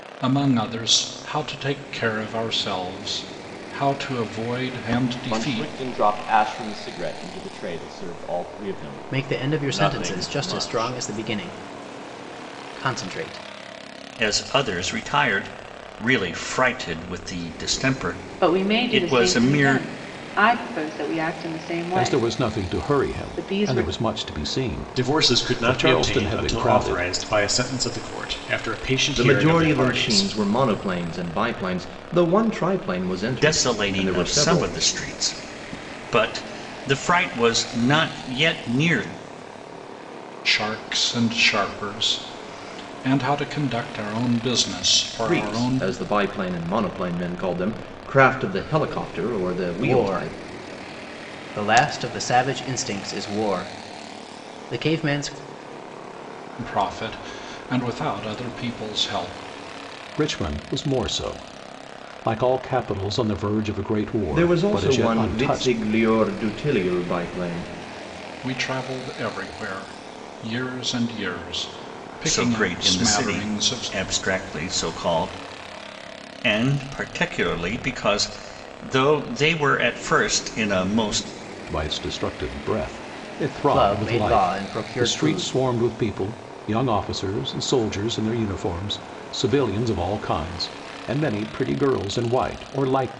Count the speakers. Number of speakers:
8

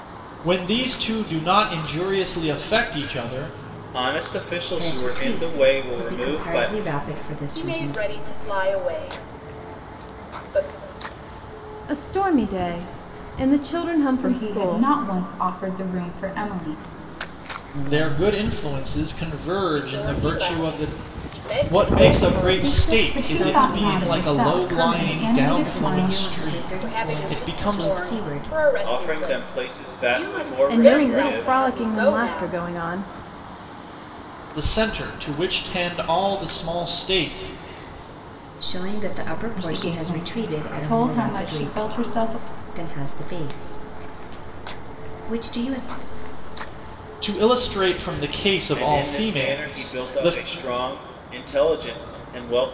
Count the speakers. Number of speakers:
6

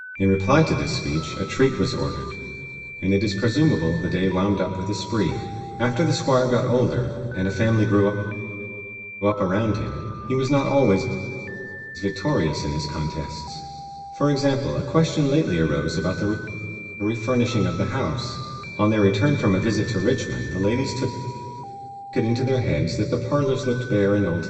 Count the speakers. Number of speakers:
1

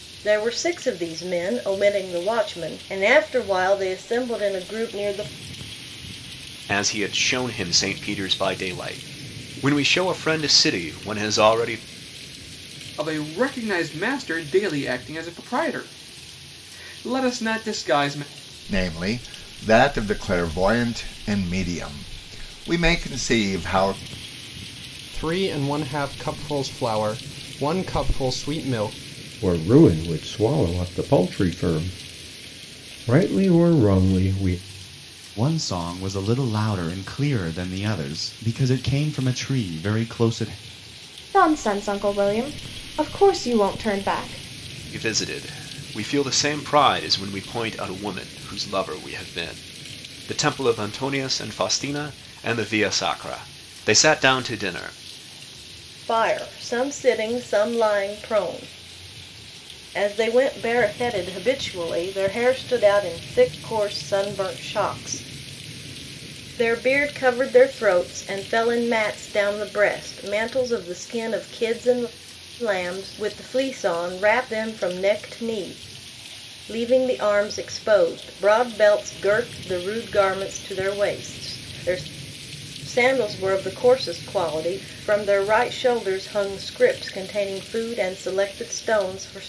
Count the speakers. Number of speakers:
8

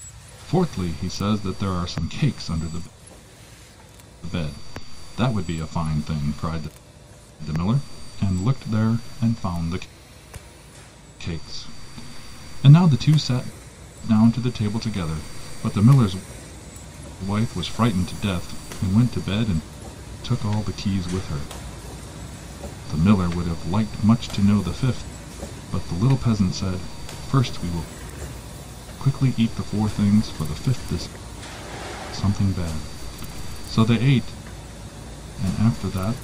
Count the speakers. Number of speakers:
1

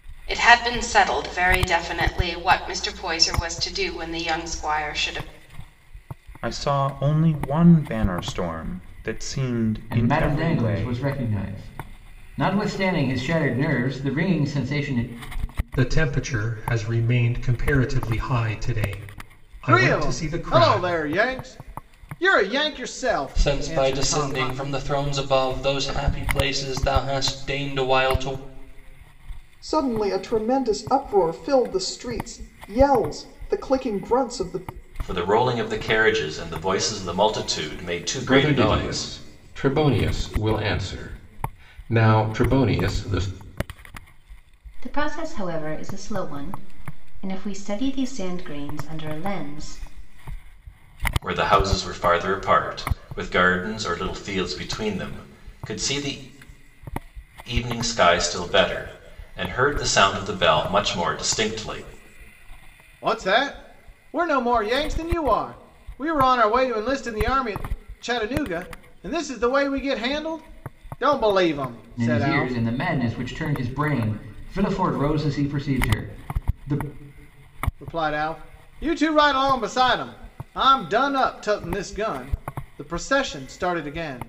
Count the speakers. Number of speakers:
10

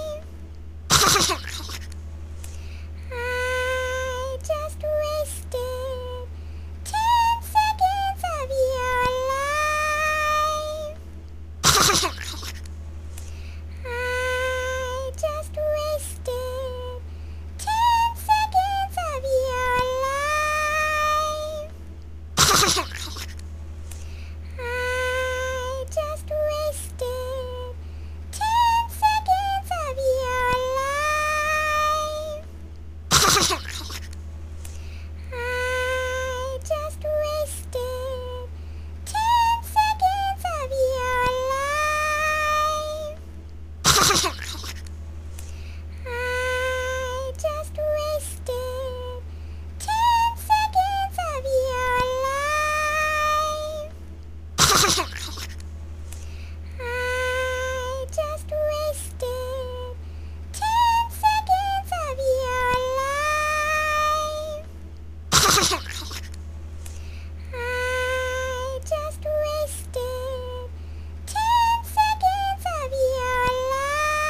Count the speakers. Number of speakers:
0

